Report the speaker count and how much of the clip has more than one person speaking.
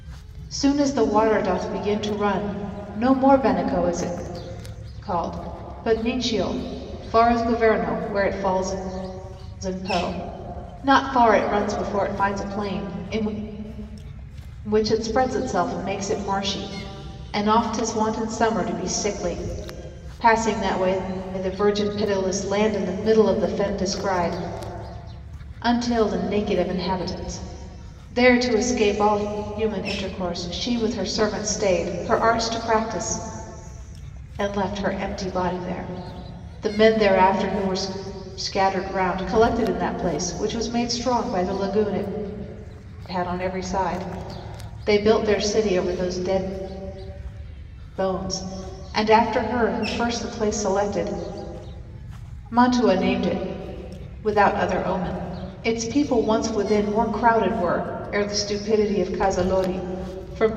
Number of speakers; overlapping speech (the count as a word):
one, no overlap